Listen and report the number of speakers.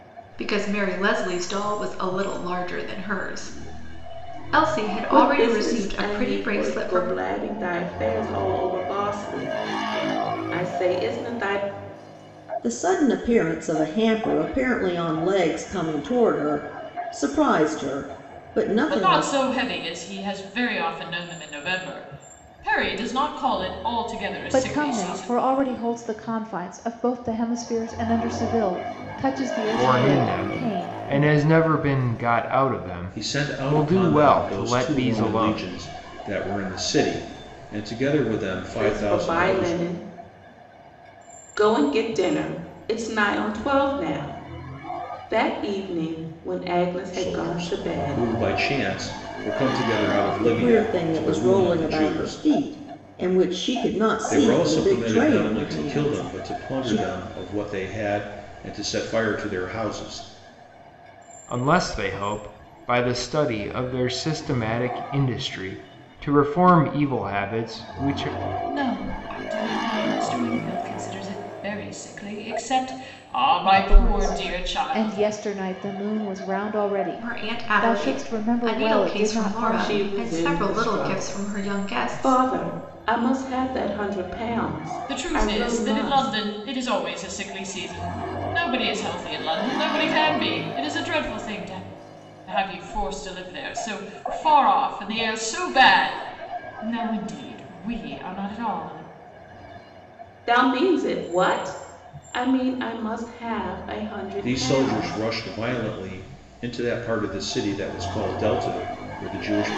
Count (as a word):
seven